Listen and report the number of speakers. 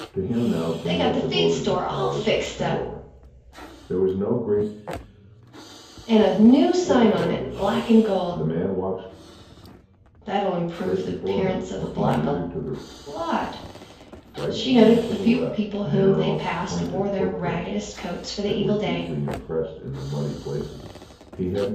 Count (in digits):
2